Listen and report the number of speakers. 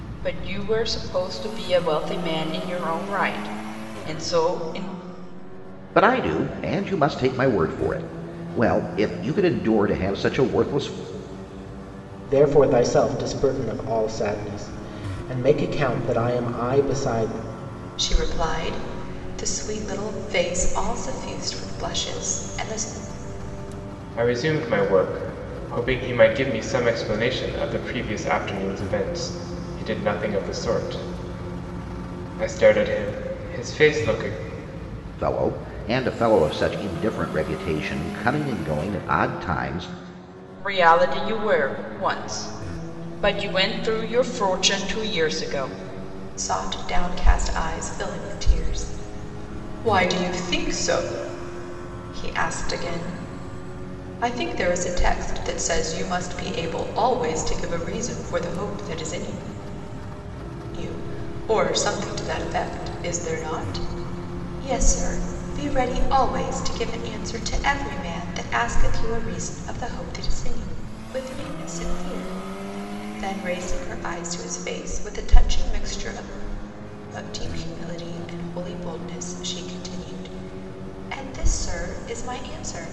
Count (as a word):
five